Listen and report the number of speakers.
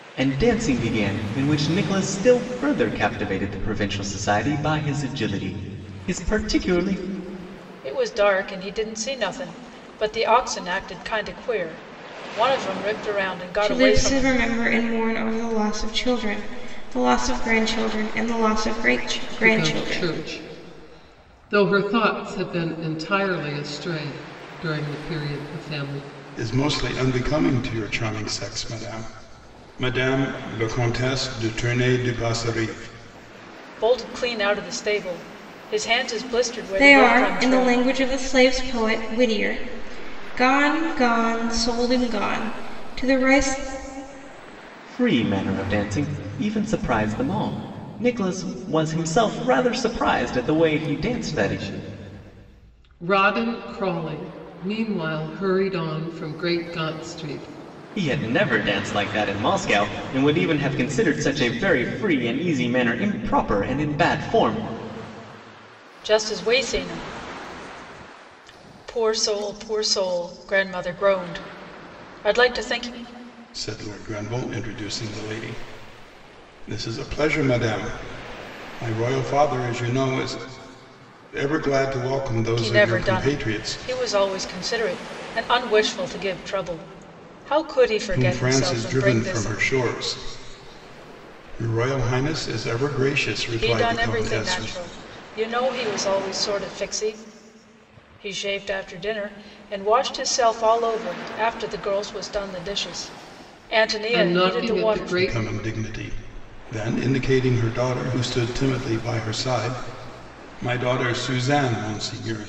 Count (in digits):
5